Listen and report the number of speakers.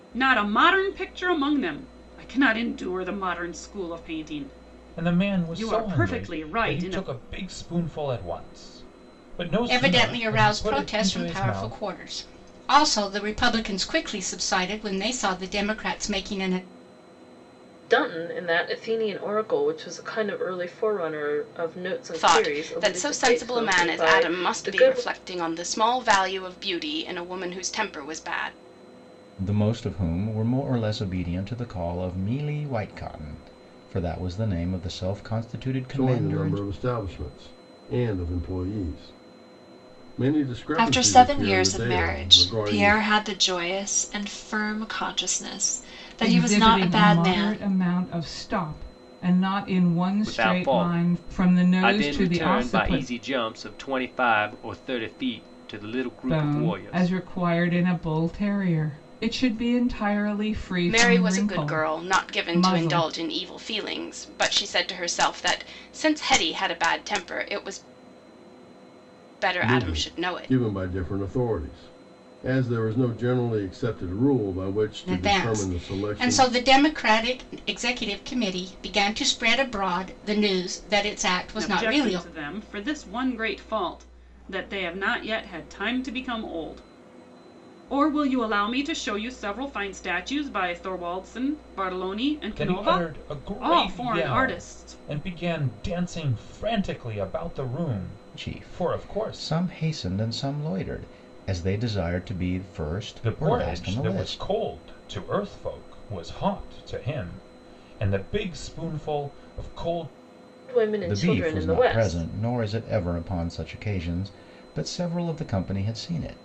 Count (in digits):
10